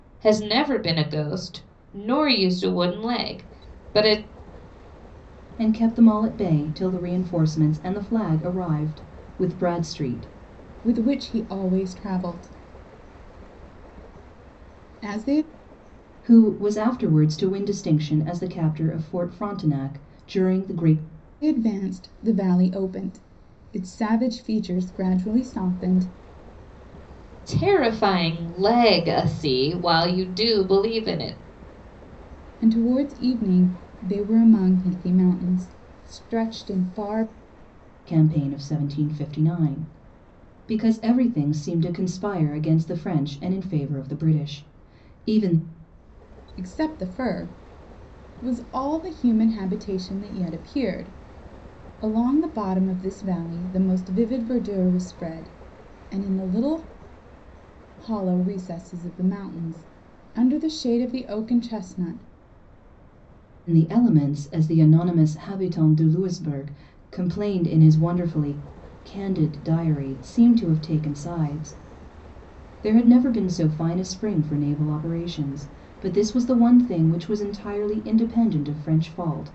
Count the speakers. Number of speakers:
three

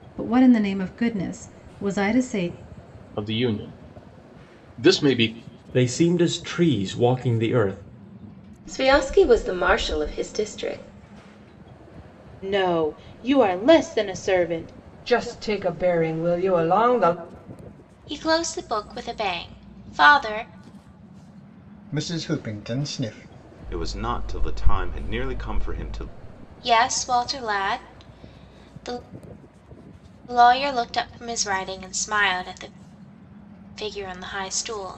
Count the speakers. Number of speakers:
nine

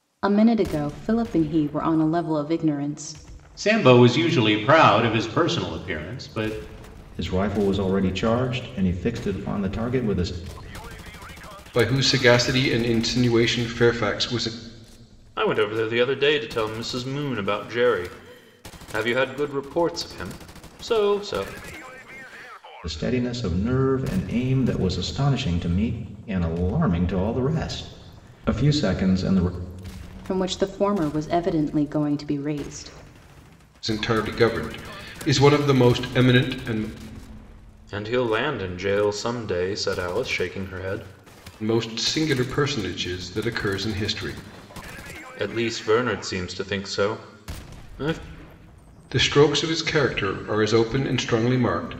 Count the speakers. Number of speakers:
five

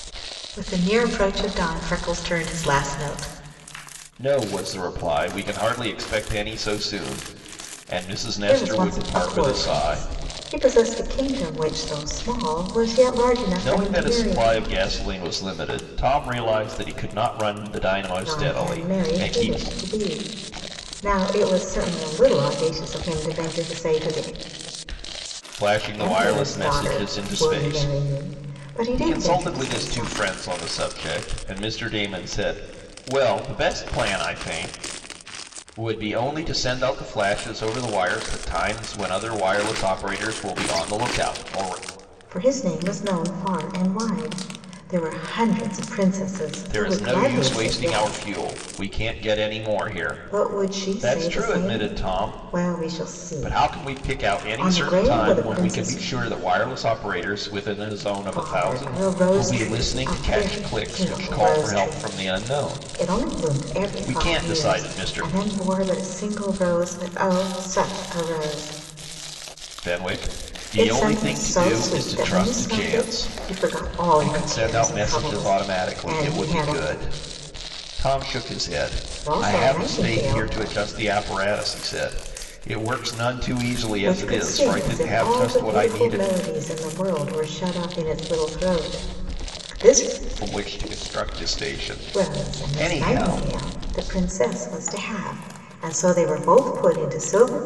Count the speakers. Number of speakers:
two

